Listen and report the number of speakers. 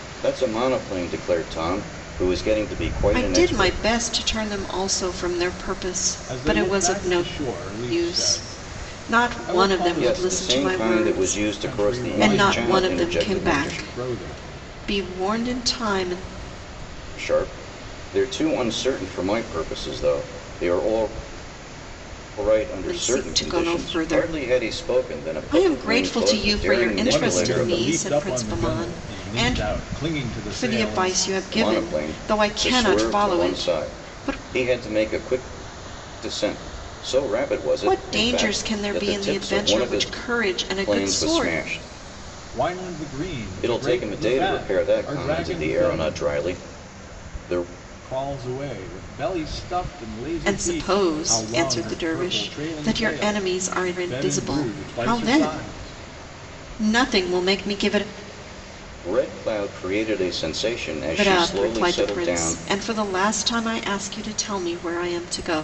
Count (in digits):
3